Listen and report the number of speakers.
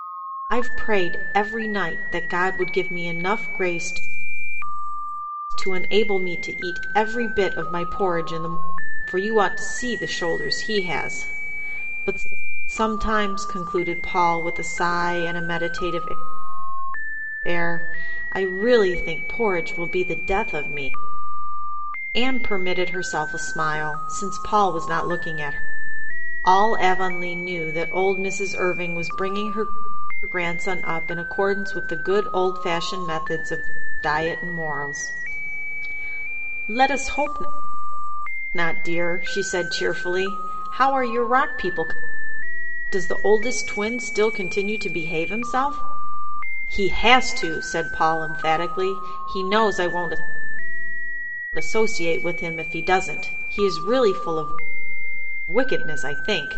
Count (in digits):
1